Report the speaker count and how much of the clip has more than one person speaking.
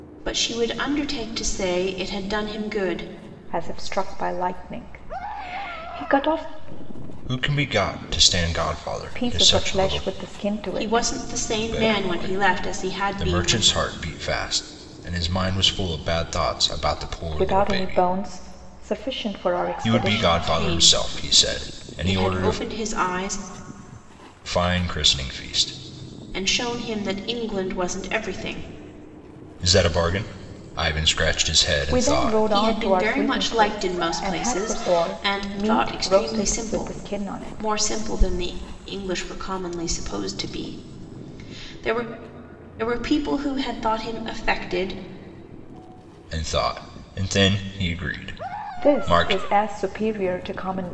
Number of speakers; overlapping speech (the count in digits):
3, about 28%